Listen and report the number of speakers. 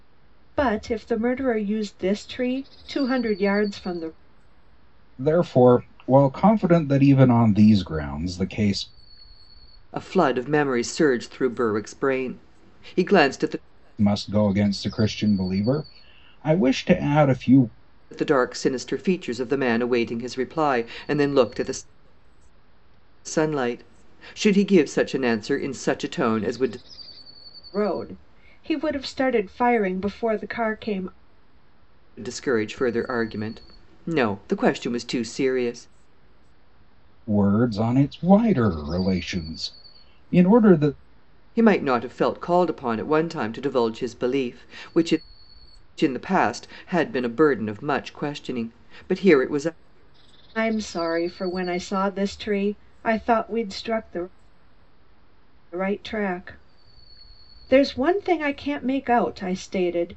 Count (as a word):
three